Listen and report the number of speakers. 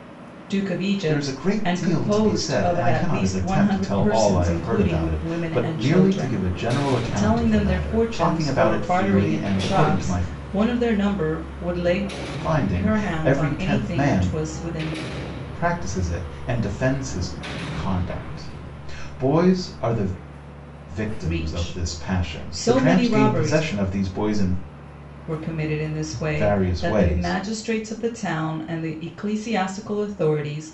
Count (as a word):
two